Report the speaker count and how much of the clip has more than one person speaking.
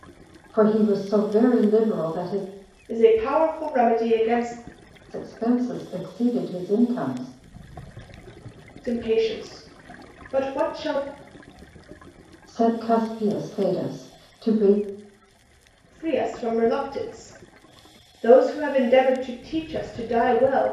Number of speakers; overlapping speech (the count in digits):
2, no overlap